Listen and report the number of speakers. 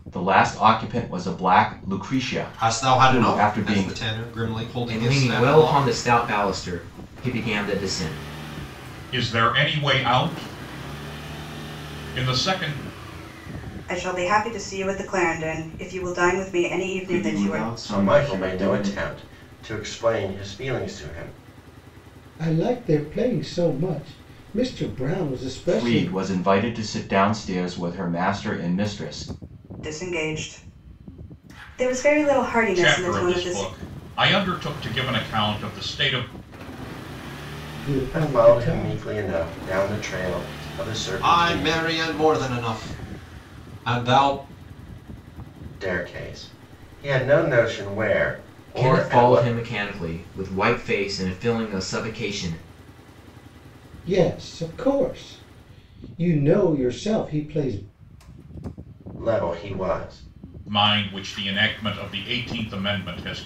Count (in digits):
8